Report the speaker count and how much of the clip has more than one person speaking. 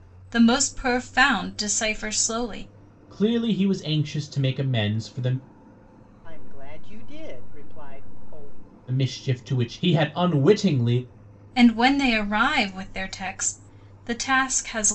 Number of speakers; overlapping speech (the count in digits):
3, no overlap